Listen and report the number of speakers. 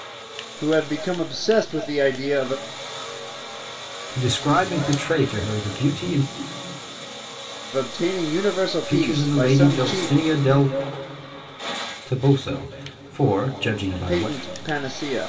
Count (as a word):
two